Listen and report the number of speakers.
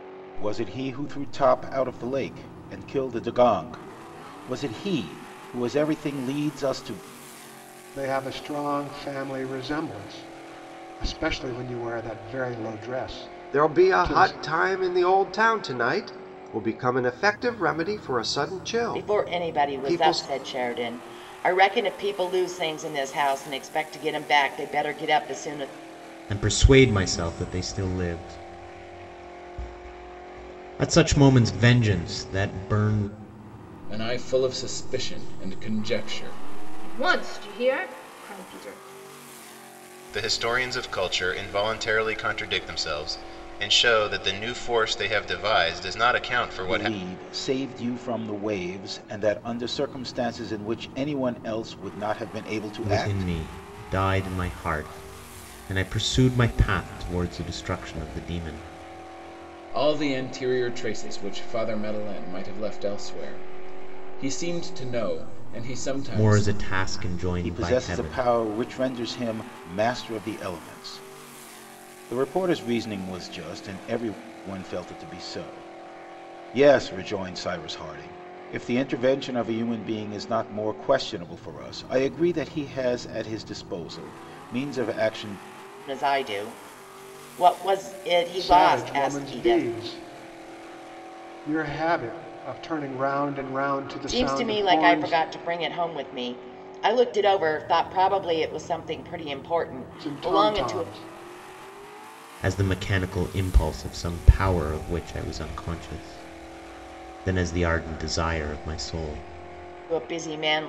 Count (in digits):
8